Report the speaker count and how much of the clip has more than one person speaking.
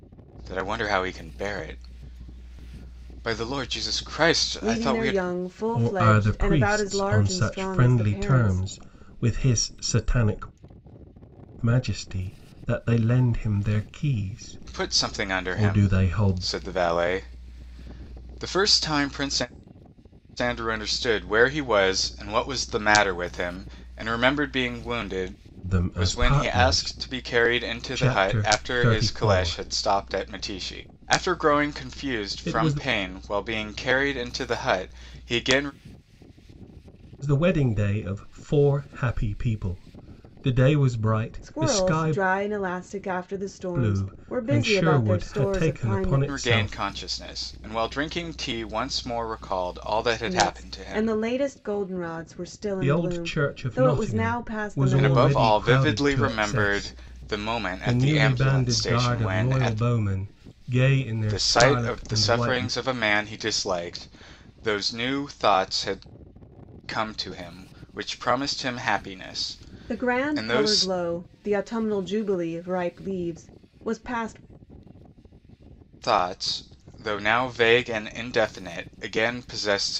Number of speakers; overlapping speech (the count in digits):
3, about 31%